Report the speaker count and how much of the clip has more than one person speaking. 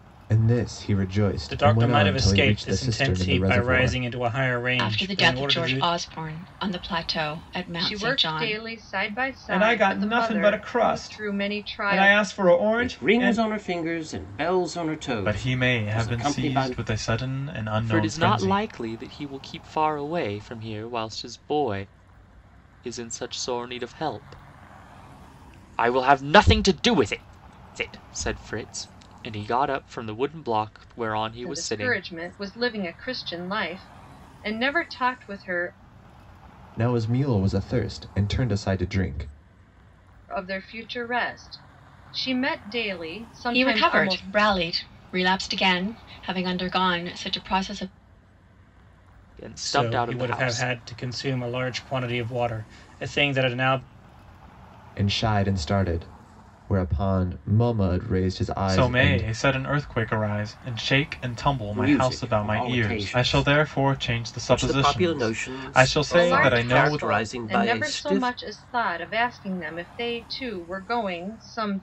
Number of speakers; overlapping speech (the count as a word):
eight, about 27%